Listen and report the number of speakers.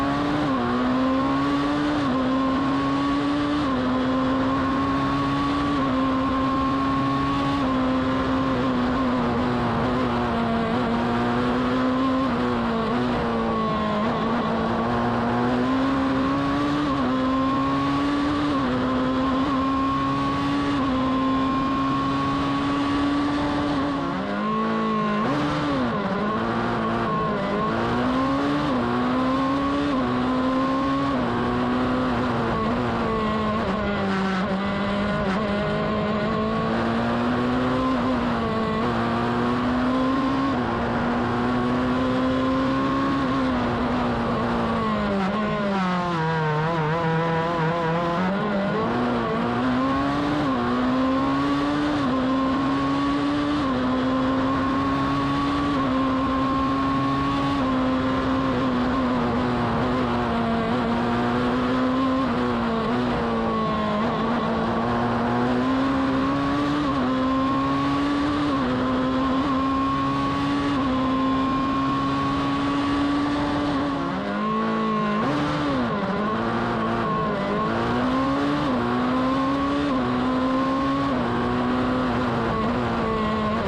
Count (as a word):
zero